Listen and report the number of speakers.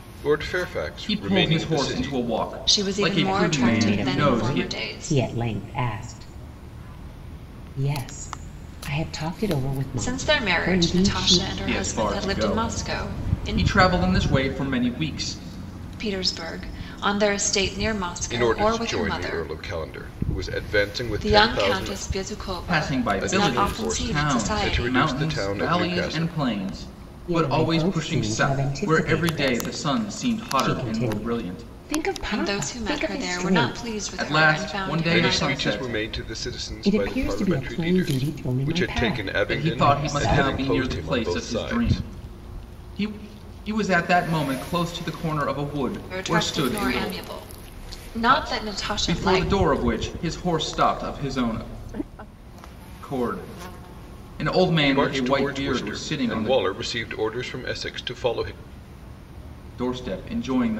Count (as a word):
four